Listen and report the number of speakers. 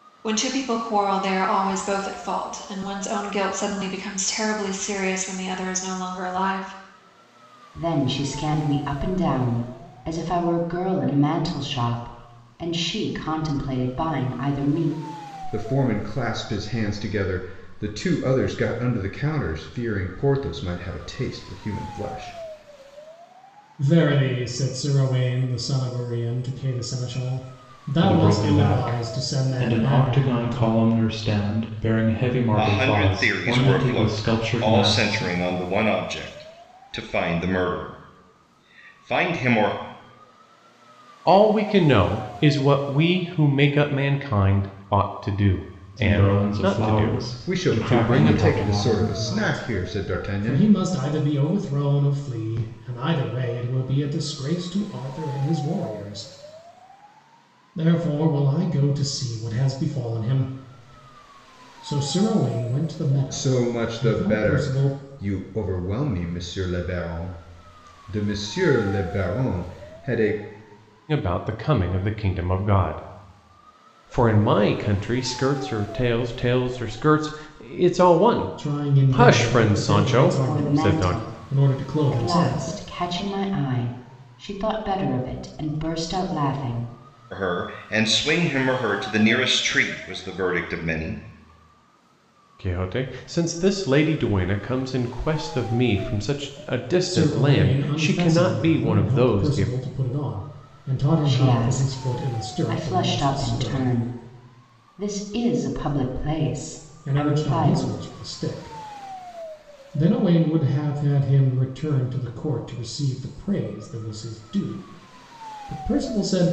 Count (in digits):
7